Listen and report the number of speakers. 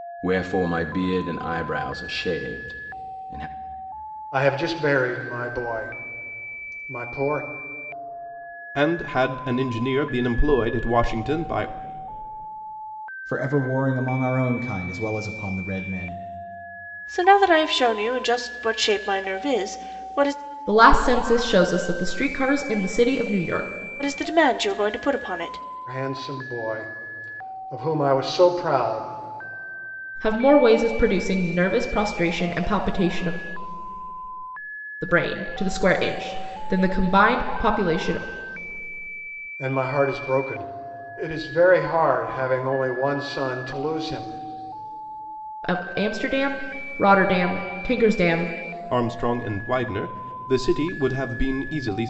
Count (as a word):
six